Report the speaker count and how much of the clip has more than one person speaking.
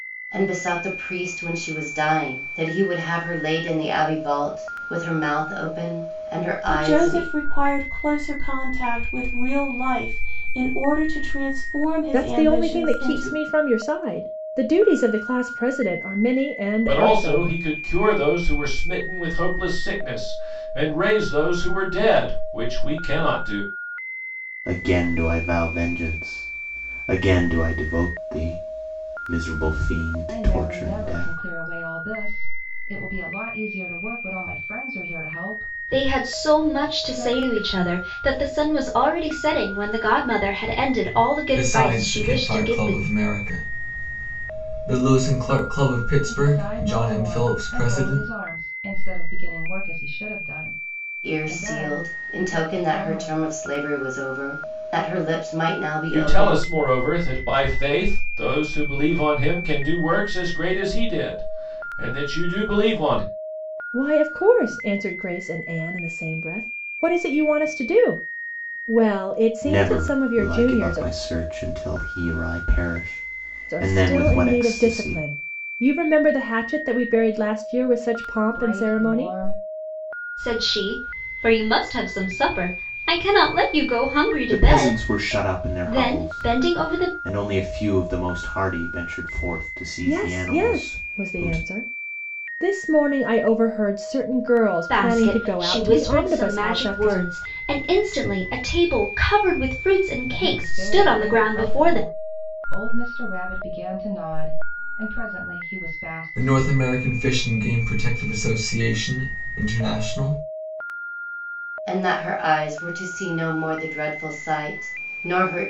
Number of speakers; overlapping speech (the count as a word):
eight, about 21%